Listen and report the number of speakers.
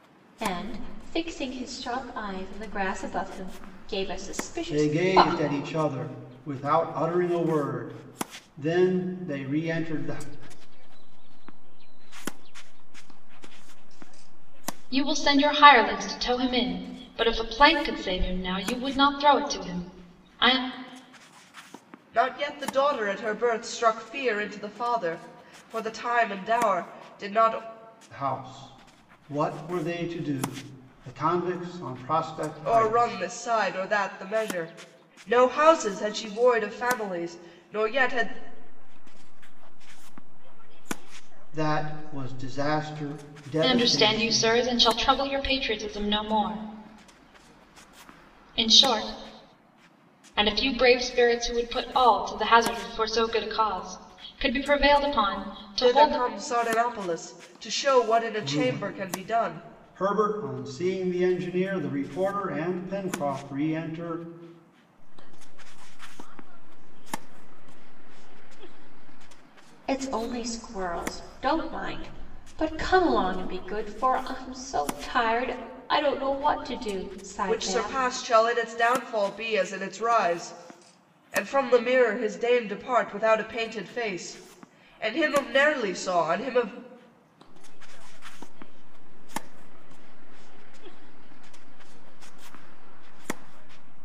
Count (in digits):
5